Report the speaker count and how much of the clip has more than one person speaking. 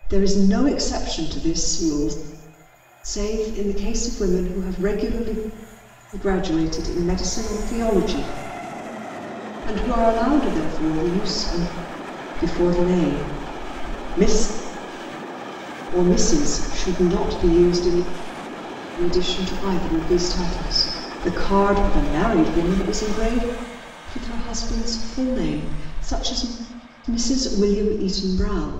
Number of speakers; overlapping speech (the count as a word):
one, no overlap